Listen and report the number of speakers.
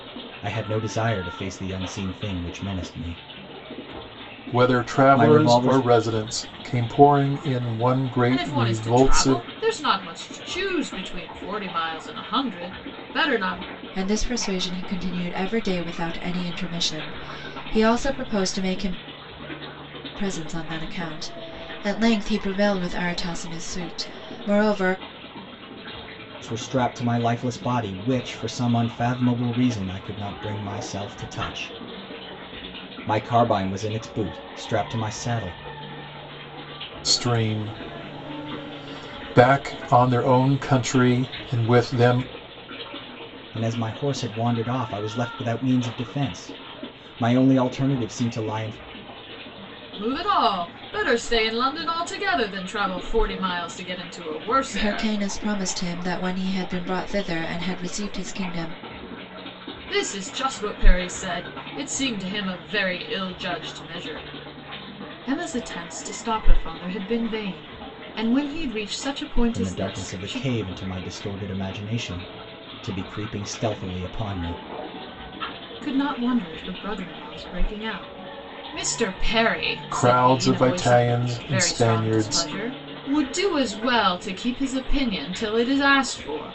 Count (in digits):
4